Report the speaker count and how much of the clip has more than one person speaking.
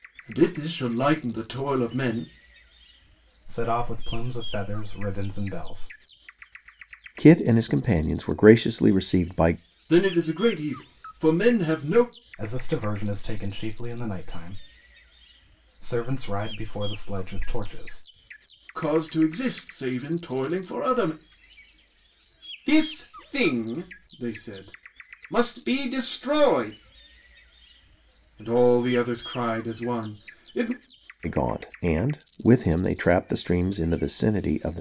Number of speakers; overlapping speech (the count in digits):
3, no overlap